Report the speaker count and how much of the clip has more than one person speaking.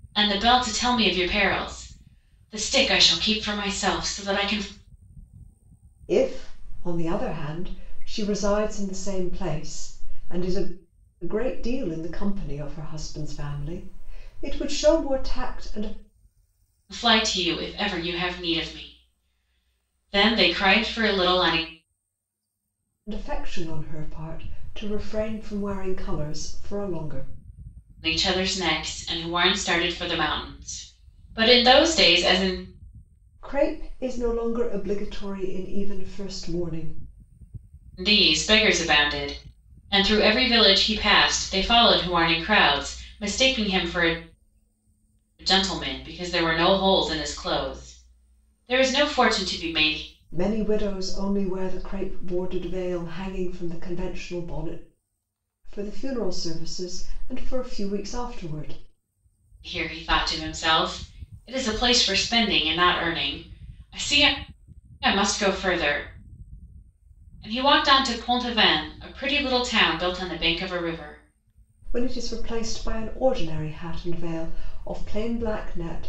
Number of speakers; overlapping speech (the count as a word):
two, no overlap